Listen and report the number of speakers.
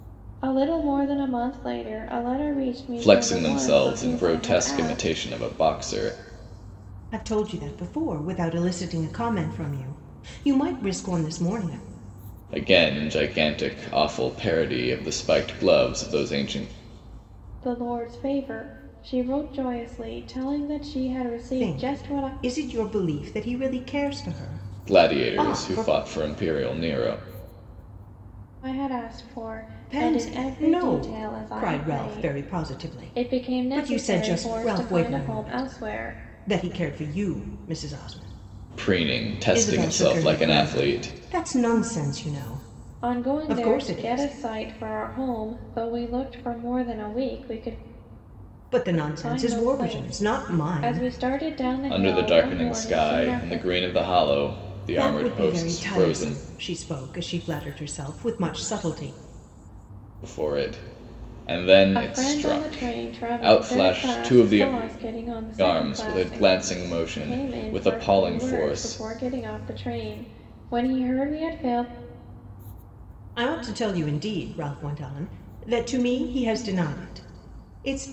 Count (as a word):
three